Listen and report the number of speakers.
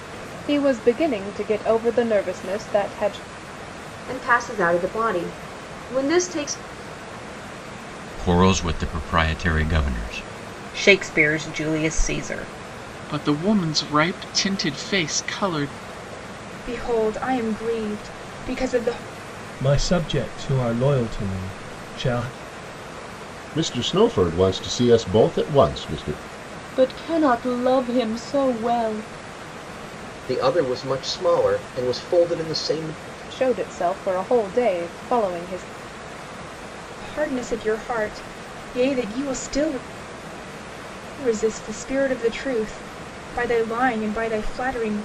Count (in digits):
10